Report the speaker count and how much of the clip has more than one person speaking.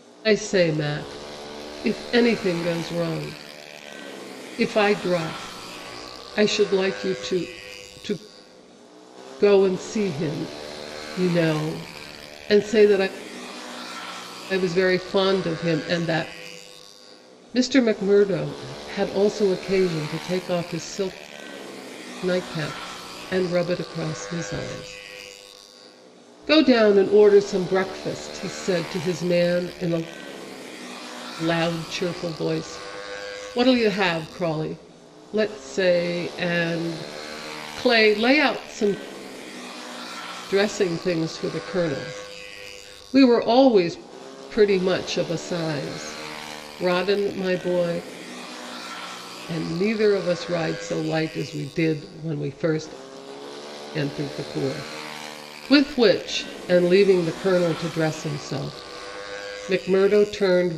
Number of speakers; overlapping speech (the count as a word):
one, no overlap